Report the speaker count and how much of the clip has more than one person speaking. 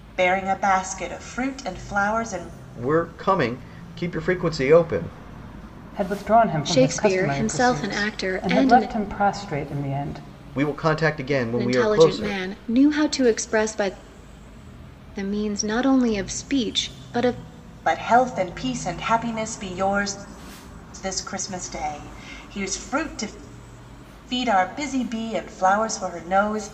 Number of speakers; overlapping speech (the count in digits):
4, about 11%